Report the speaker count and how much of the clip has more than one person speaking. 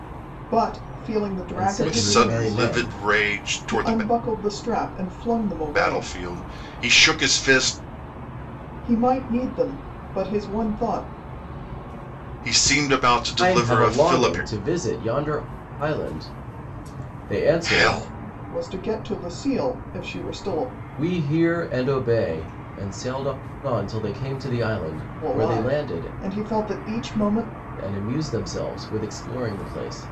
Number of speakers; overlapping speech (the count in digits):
3, about 16%